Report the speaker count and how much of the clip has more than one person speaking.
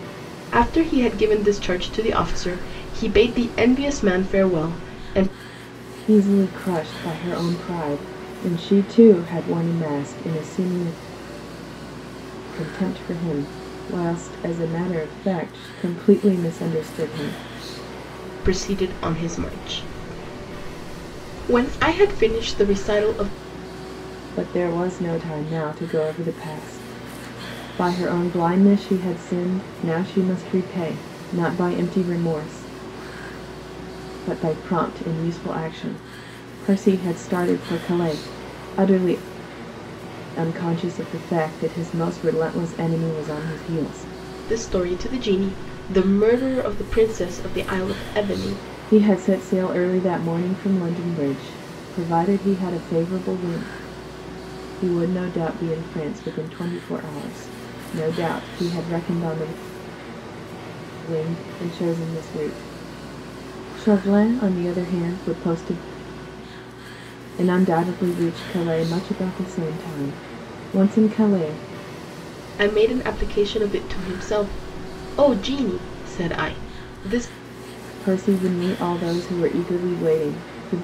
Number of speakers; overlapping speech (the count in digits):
2, no overlap